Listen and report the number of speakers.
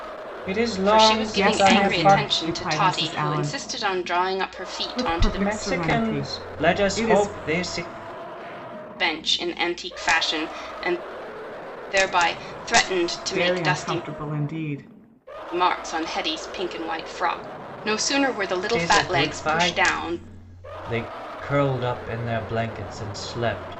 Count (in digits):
3